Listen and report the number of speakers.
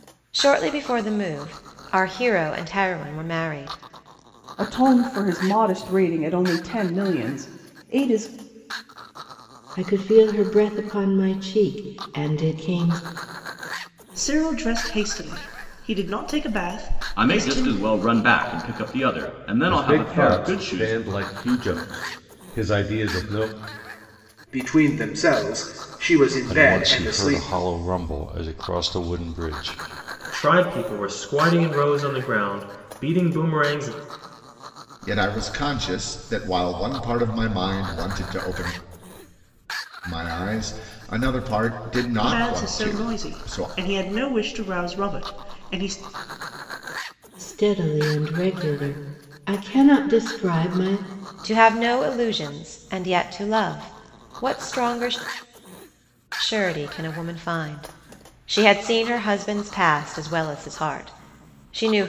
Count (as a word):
ten